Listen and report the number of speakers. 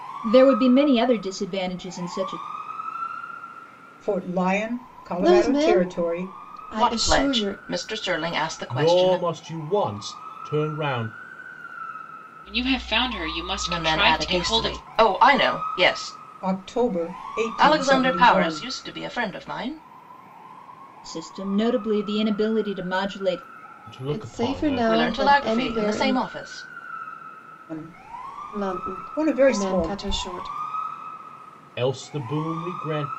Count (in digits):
6